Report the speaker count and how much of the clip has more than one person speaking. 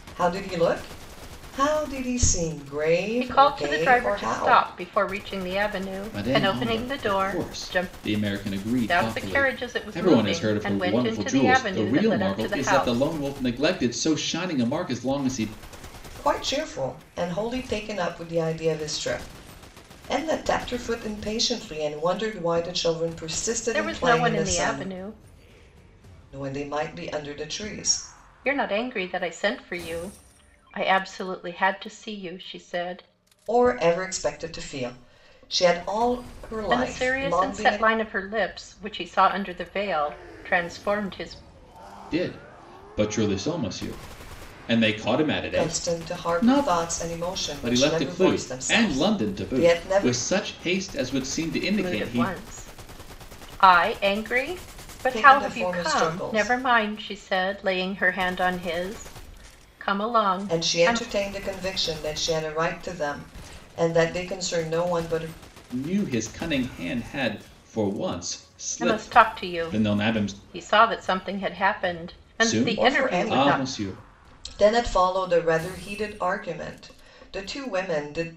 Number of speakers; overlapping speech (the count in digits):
3, about 25%